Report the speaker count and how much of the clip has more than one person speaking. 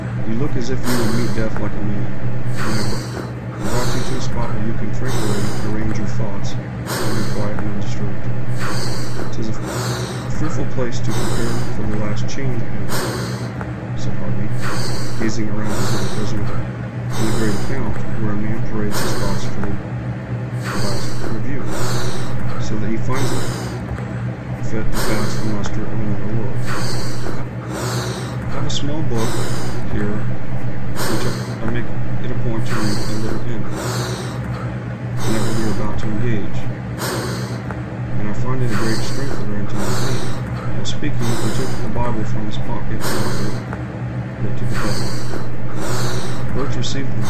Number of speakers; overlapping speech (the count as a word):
one, no overlap